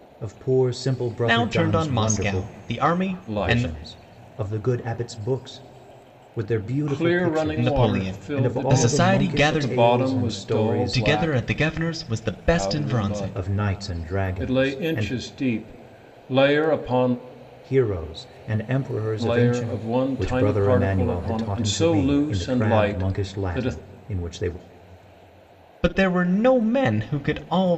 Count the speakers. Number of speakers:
3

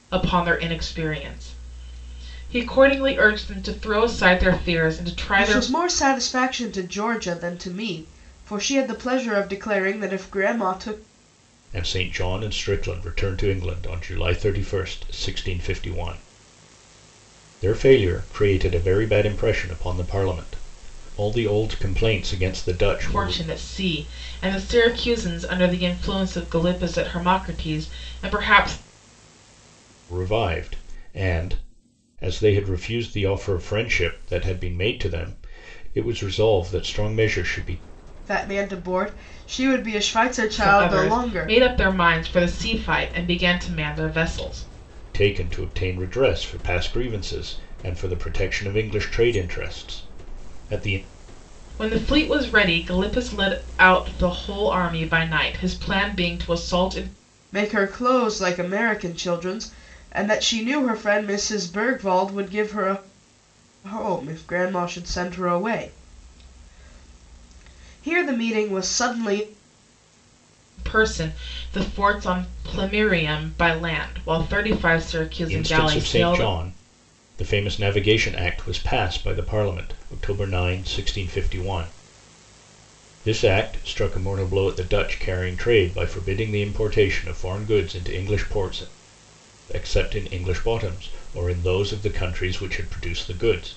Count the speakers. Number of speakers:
3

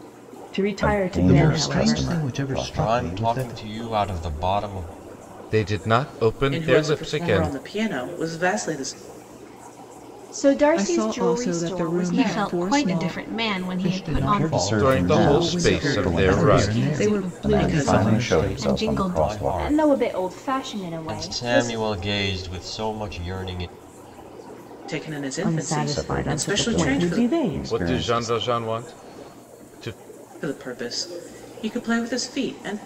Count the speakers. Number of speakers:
9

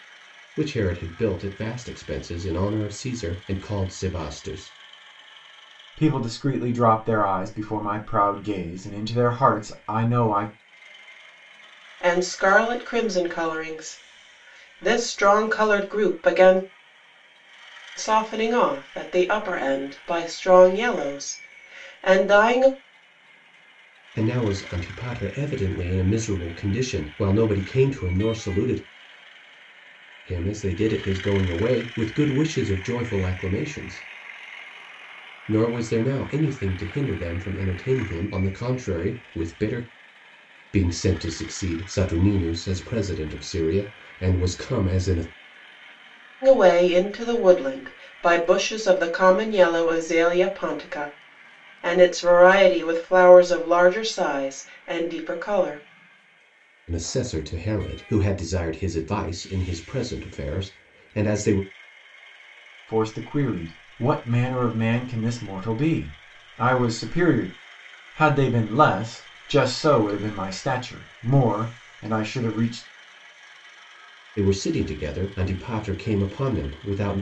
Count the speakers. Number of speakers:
3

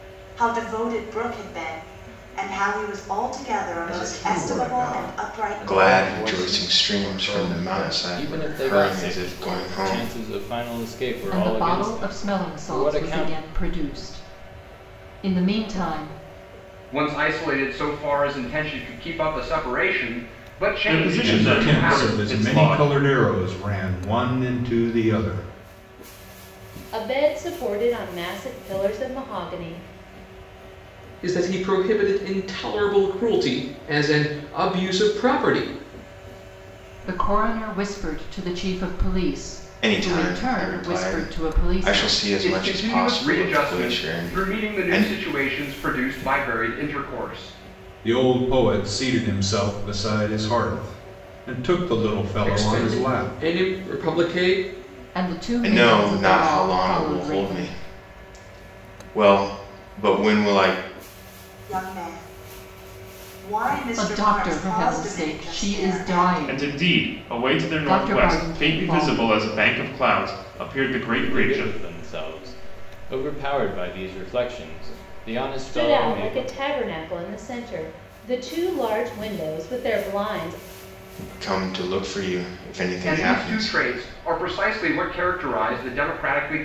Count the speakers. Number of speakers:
10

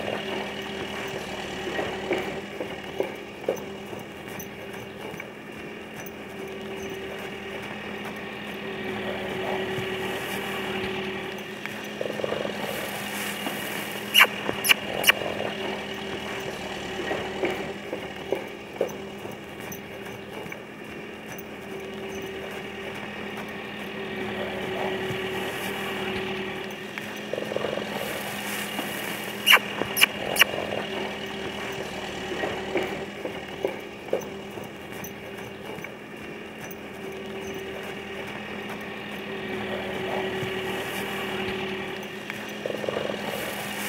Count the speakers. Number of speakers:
0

